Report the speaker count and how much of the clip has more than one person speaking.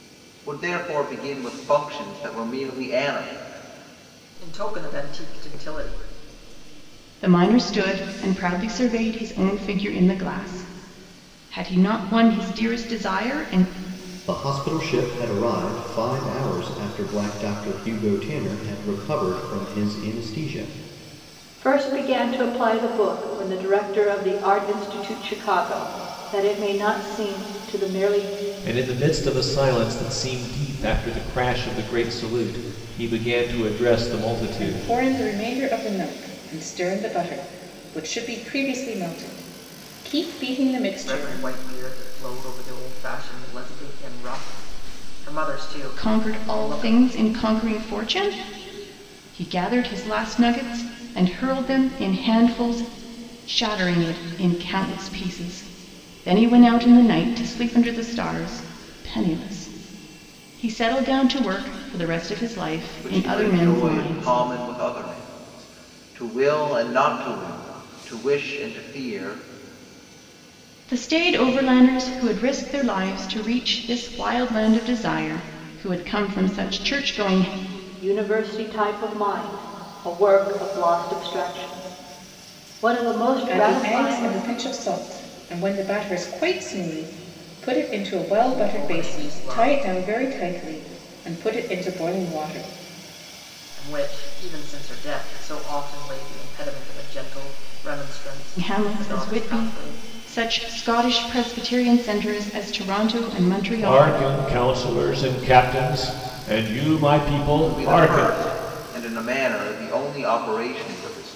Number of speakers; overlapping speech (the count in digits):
7, about 8%